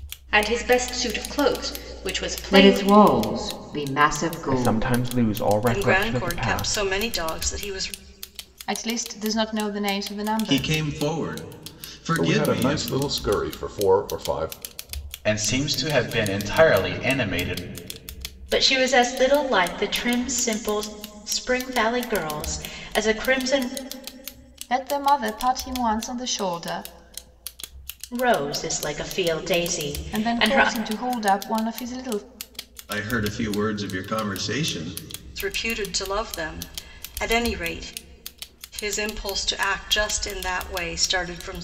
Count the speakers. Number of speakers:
9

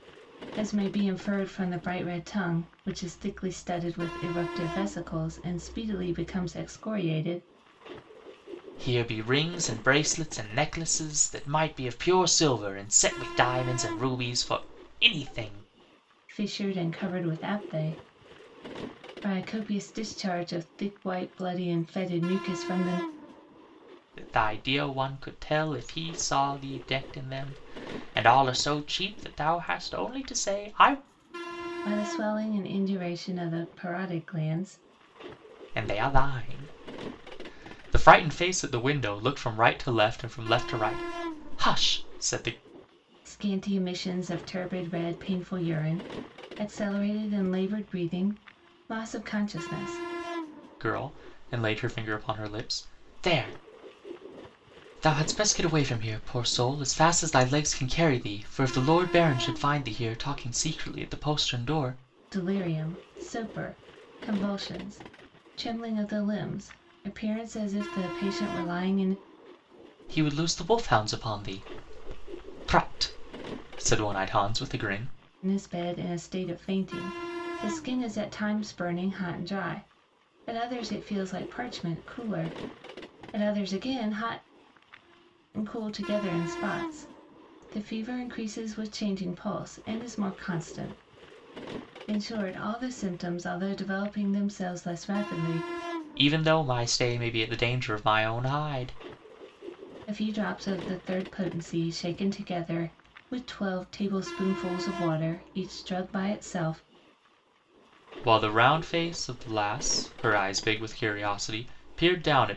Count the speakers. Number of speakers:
2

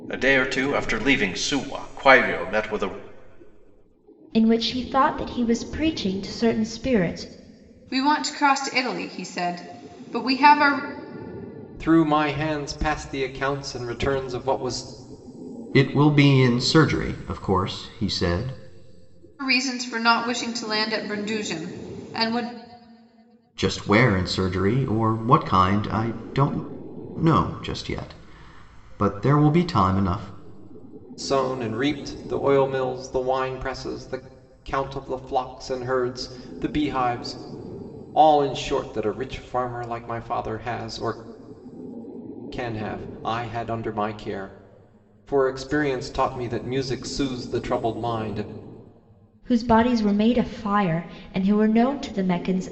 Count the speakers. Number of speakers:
5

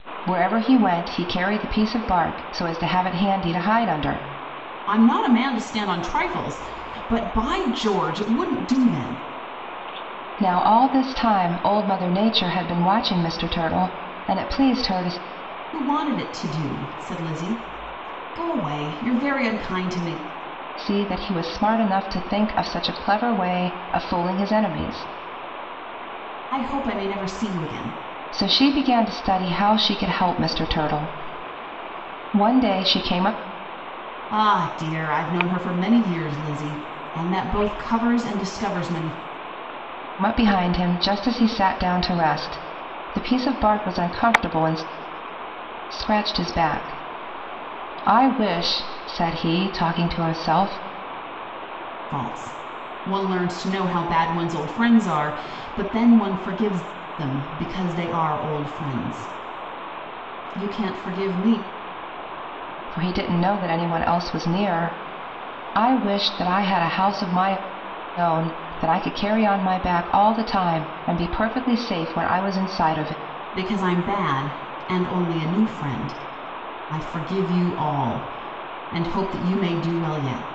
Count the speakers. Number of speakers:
2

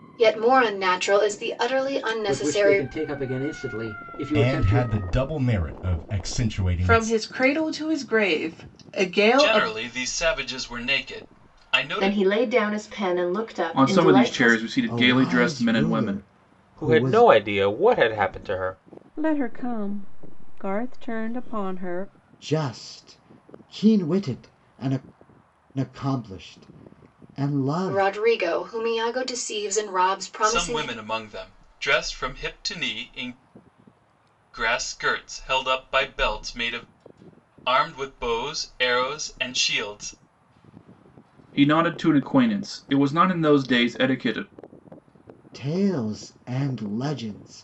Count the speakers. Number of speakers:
10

